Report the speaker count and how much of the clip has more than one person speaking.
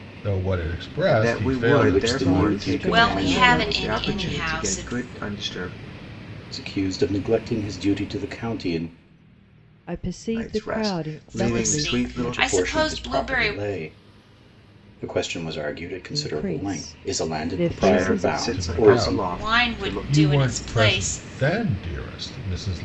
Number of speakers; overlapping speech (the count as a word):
five, about 54%